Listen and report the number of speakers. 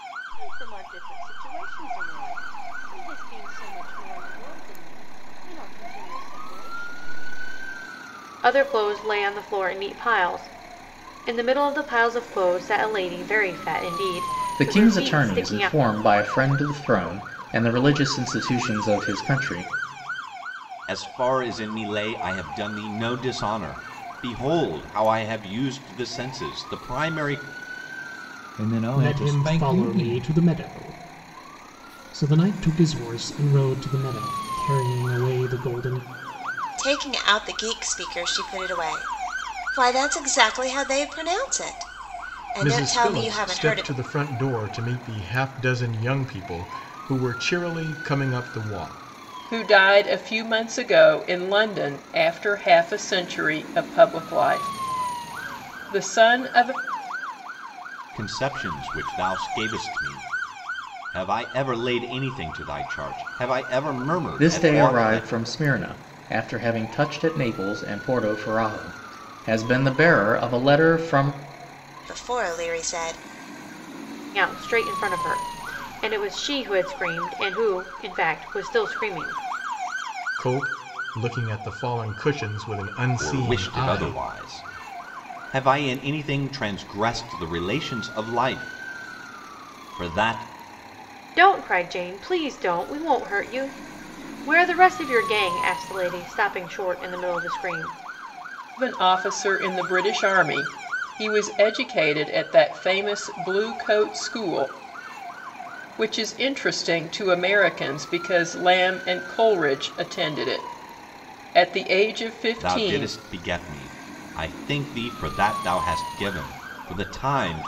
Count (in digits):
9